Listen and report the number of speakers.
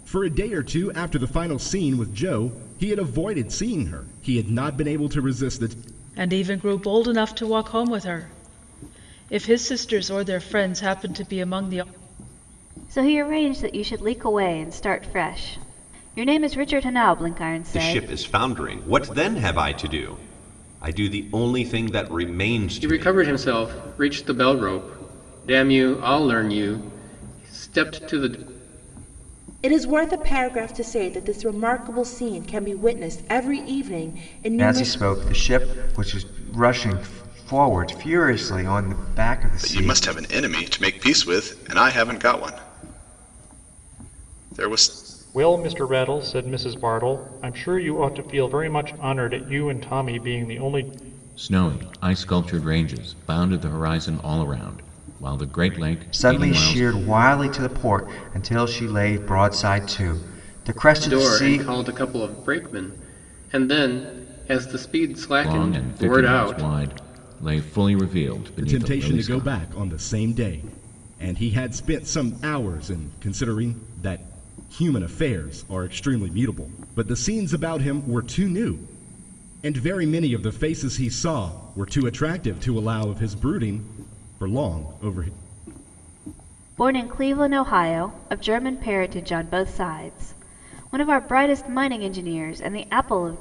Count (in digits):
10